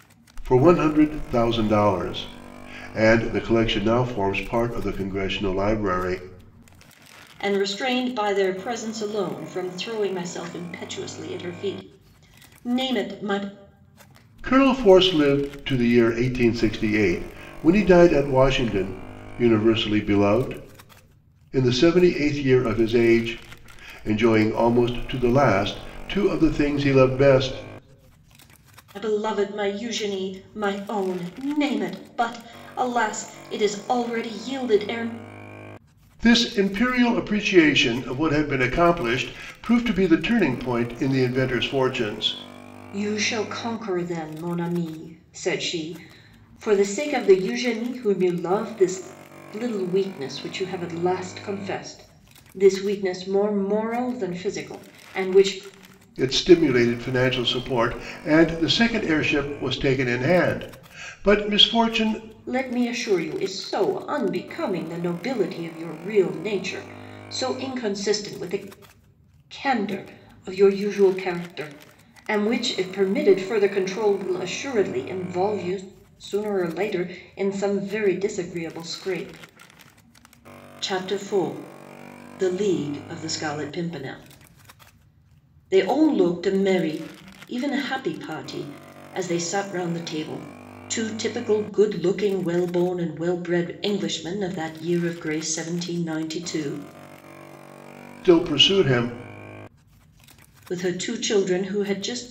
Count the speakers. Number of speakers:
2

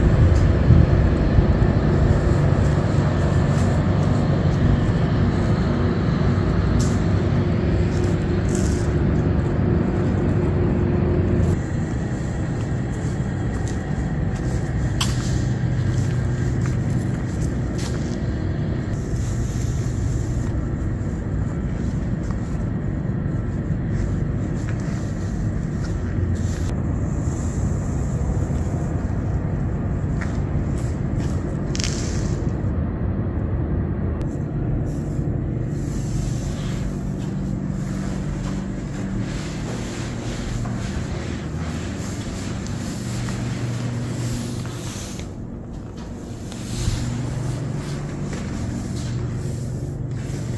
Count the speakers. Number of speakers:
0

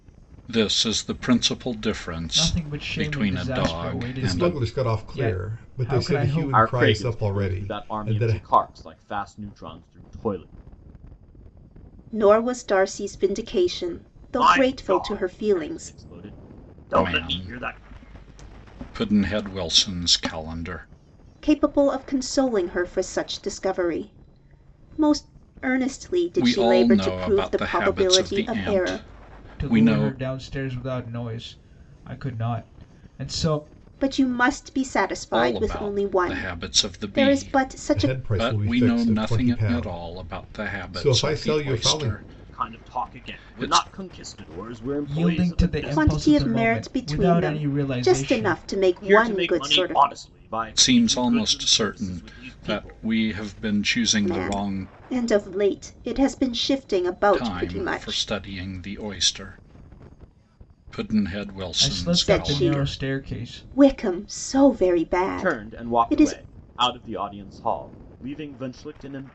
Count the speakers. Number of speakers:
5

